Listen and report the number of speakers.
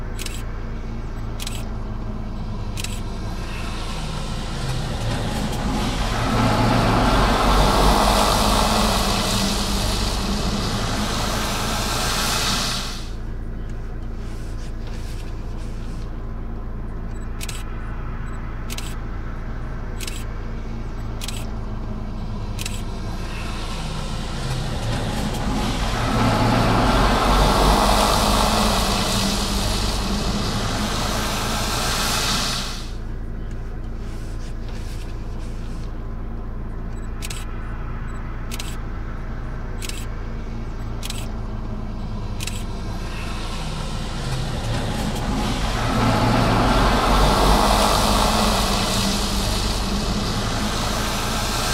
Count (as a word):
zero